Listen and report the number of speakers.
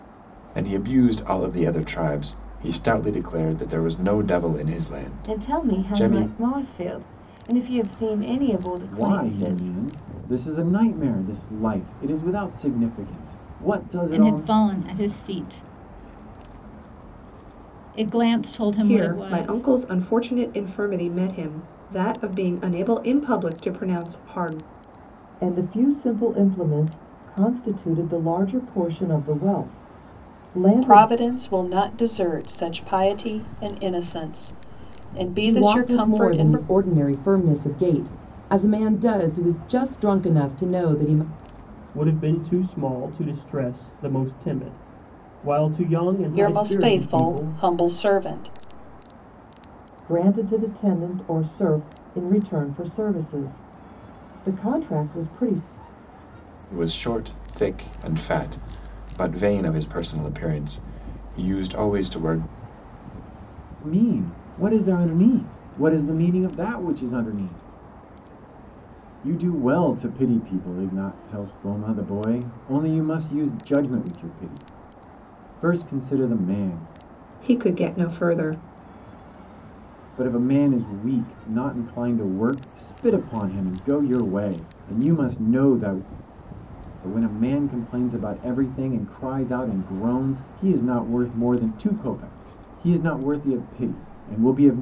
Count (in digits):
9